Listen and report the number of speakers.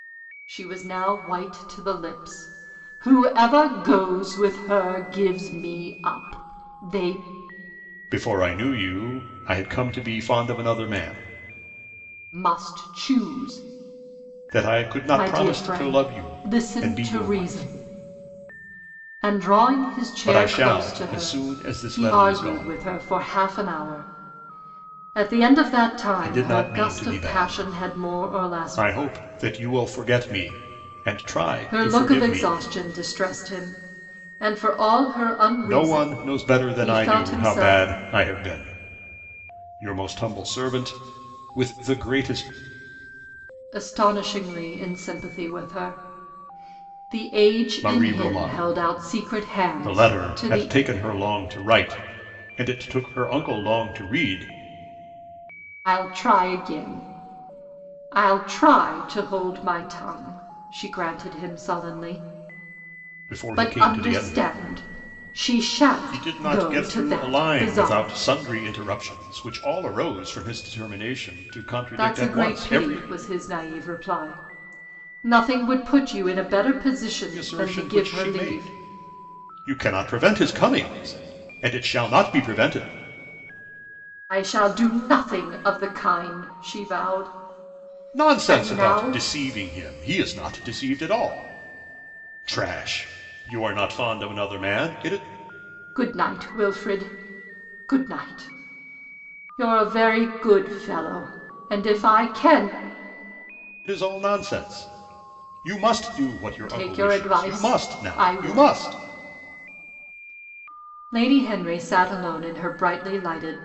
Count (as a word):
two